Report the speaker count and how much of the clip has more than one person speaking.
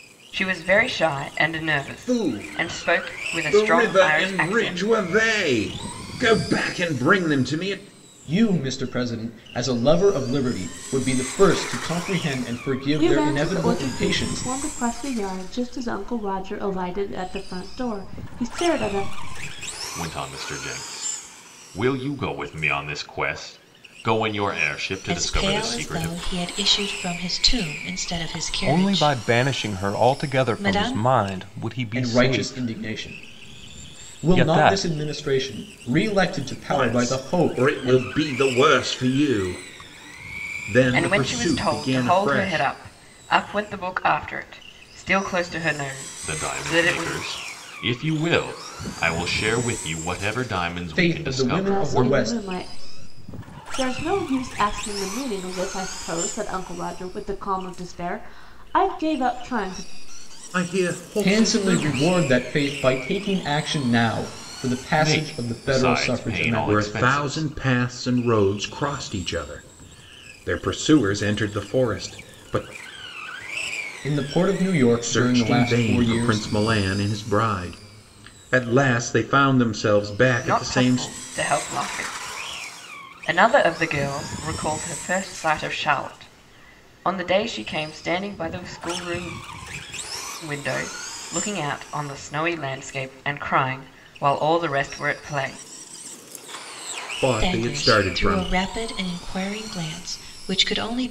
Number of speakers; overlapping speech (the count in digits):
7, about 23%